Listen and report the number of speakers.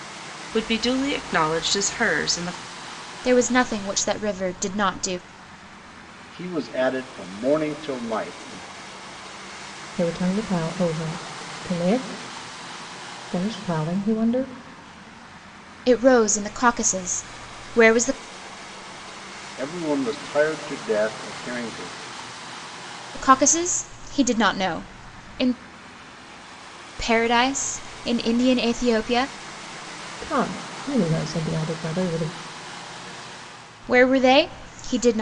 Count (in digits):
4